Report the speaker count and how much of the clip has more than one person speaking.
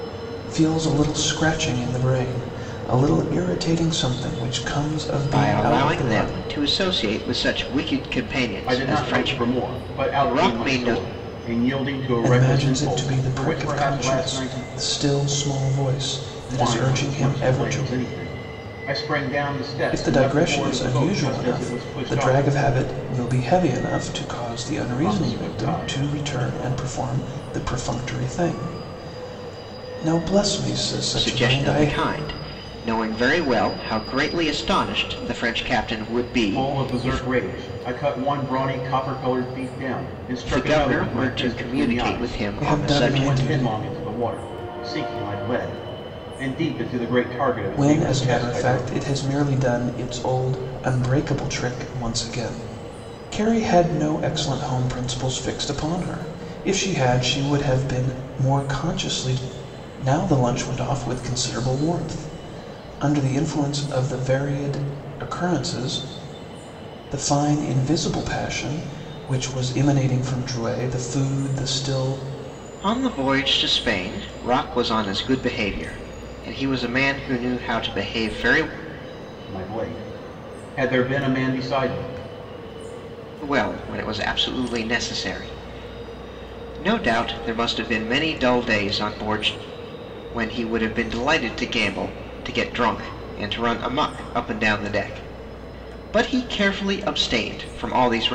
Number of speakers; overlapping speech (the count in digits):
3, about 17%